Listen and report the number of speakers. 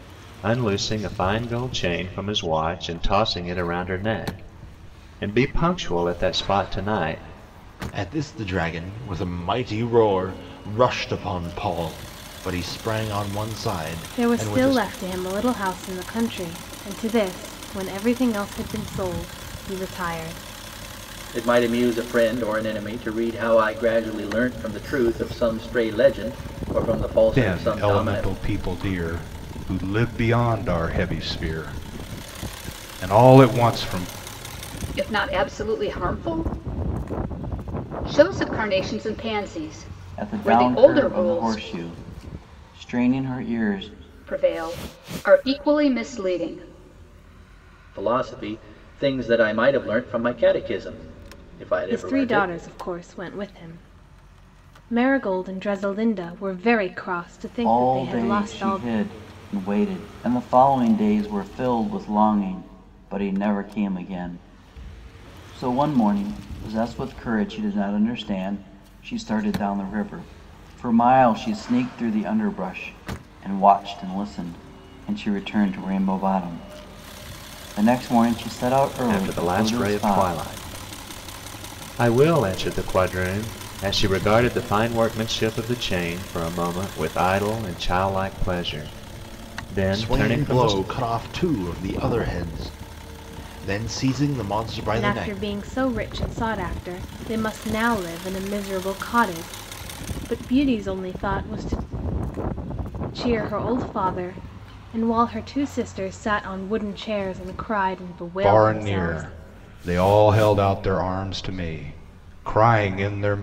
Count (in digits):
7